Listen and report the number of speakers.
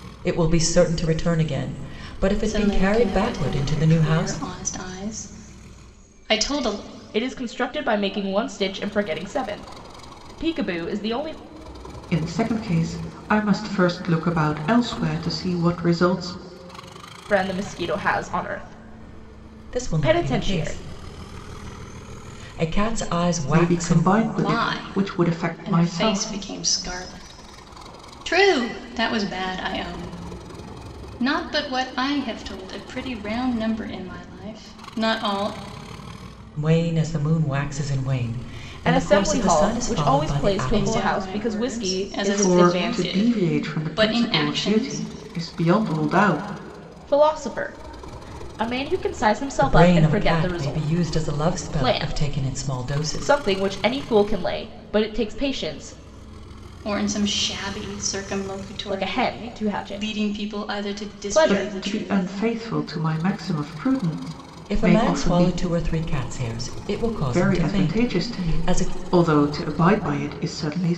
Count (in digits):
4